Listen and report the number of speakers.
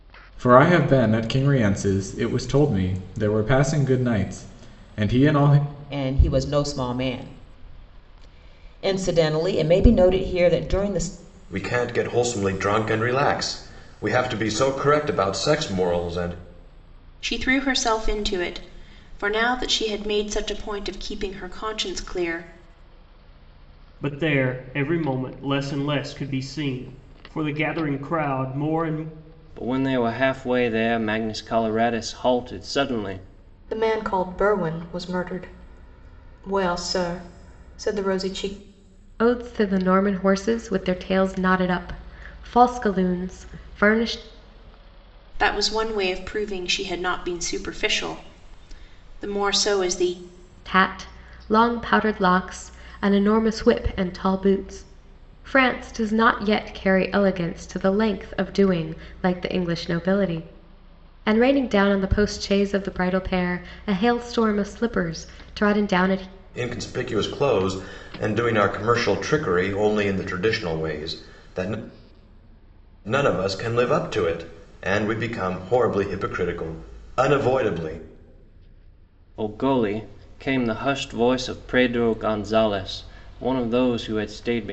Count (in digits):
8